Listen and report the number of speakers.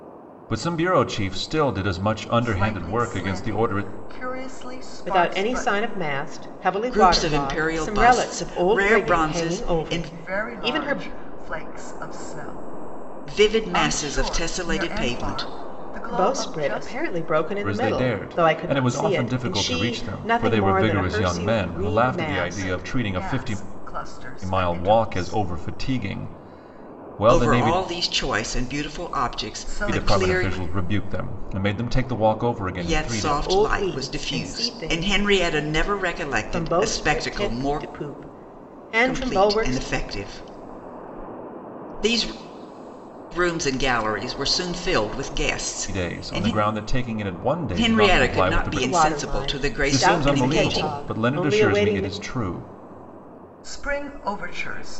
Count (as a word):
four